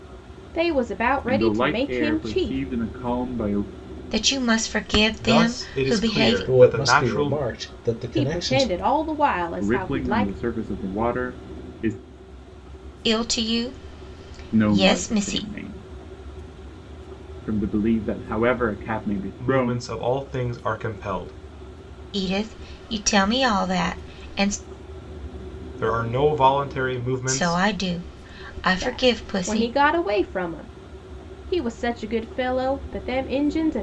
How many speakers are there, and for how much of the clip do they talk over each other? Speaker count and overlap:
five, about 23%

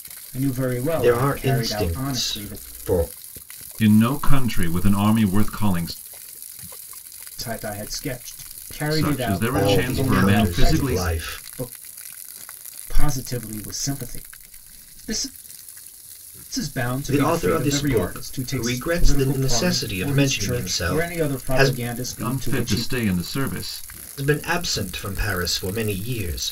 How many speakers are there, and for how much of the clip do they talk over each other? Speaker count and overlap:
three, about 37%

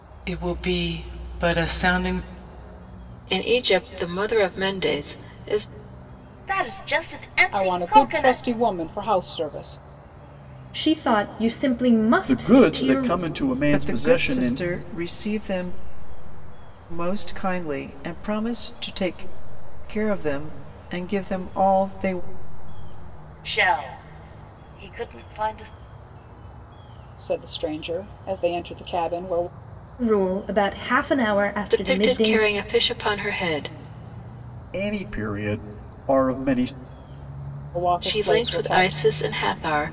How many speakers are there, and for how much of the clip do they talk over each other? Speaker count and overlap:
seven, about 12%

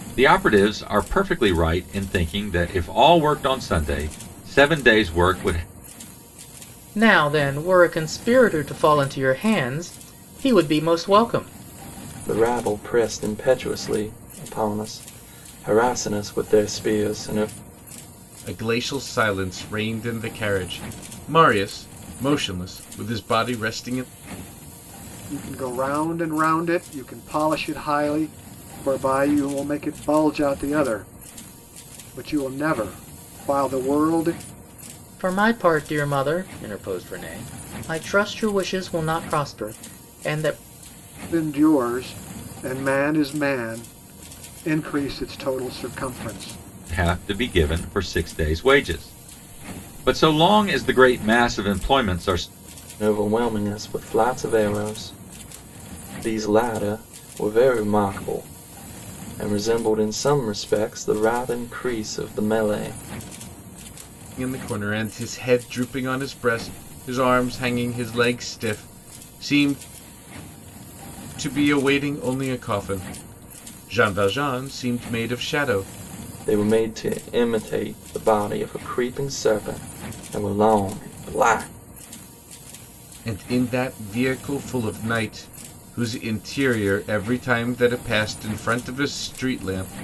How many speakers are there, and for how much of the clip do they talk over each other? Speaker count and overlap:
five, no overlap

